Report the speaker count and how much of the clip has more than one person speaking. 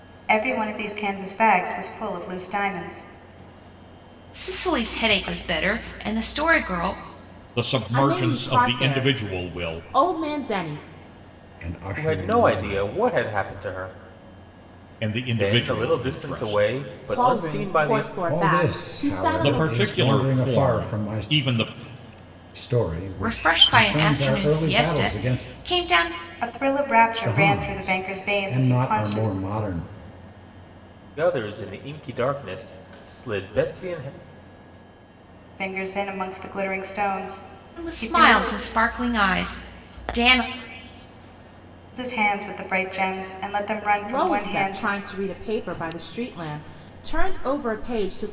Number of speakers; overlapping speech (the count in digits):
6, about 30%